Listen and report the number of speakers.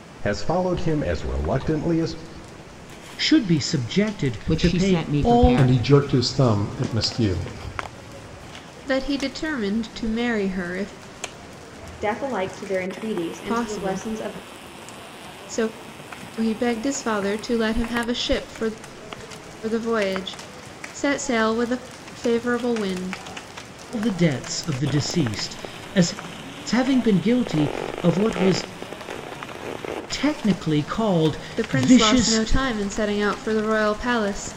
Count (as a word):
six